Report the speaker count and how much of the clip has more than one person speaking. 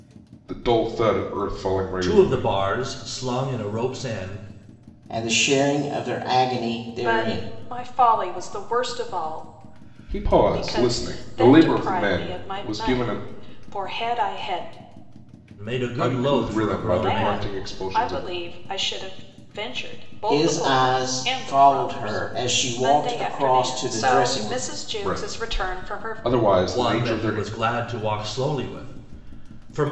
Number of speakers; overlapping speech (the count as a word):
four, about 42%